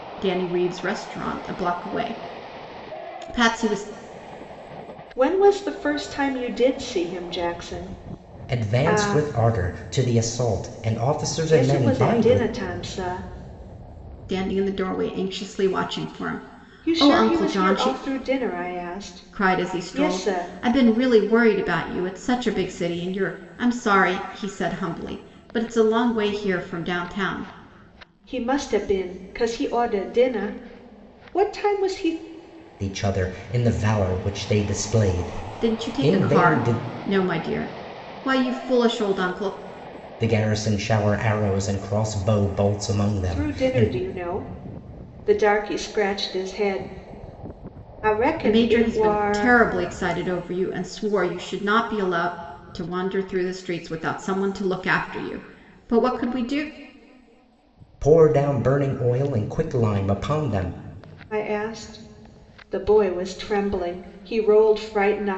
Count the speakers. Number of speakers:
3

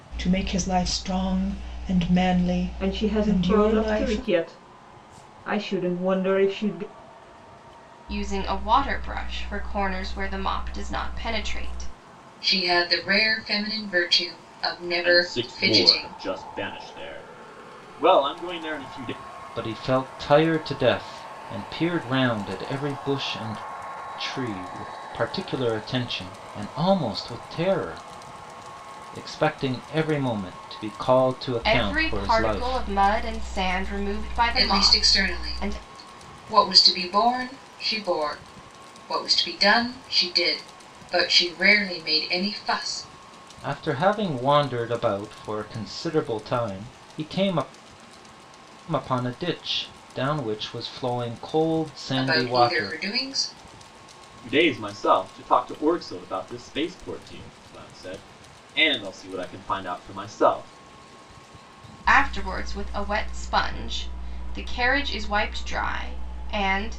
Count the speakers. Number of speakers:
6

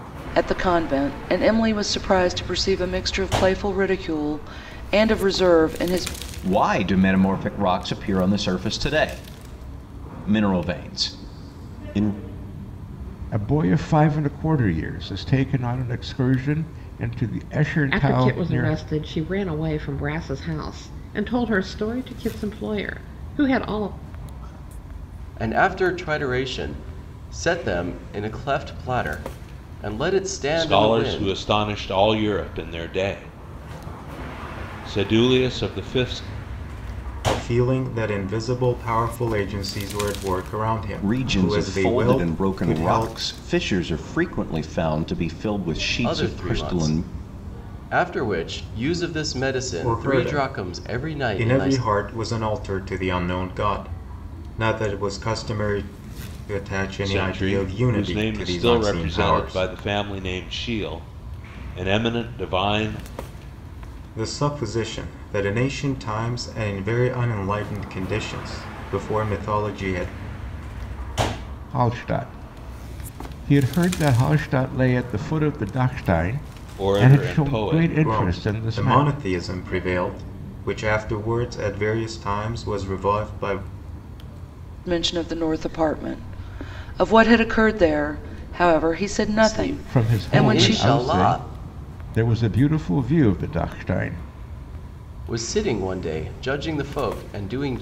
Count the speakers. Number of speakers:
7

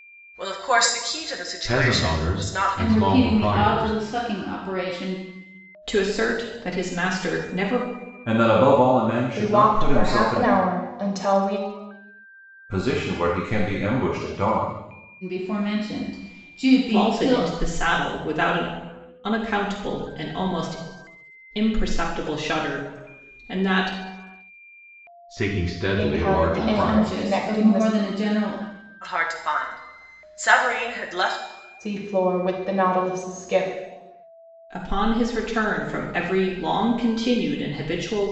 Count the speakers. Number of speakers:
6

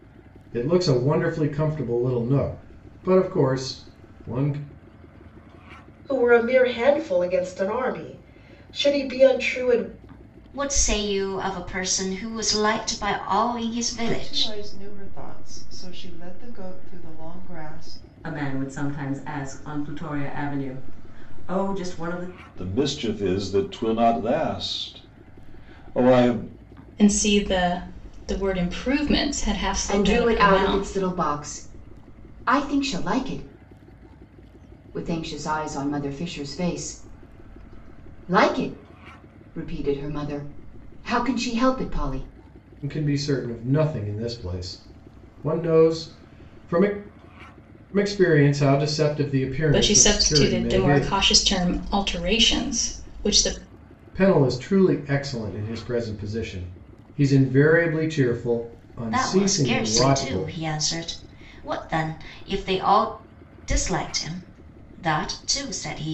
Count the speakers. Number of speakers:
8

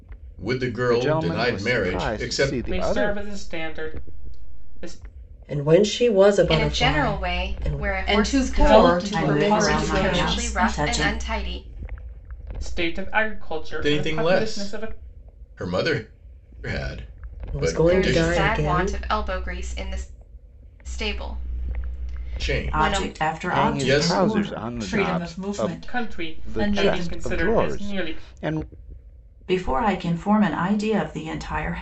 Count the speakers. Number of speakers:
8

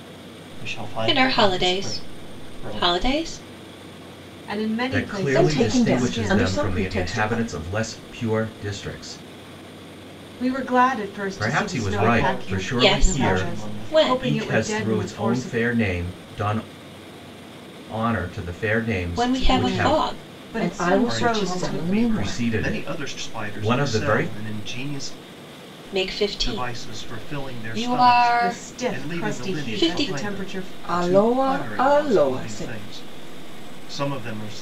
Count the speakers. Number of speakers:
5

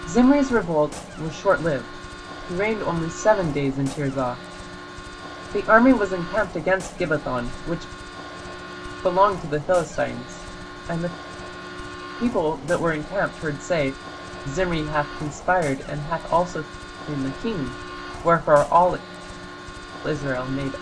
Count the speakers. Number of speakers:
1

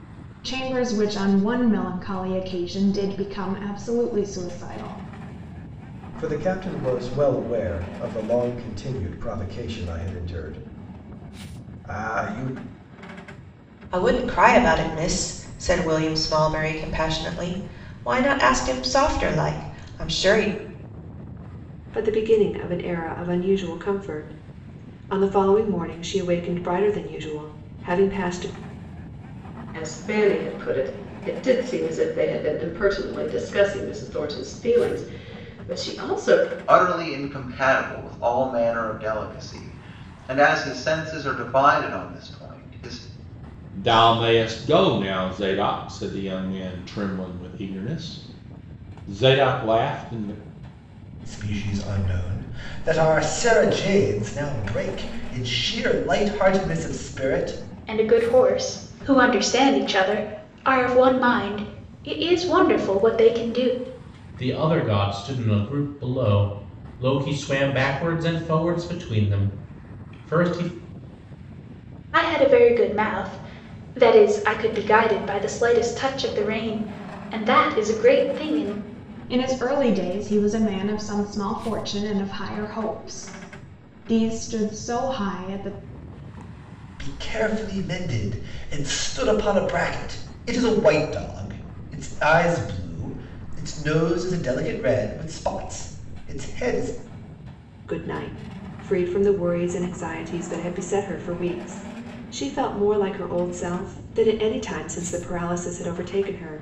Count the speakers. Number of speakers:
10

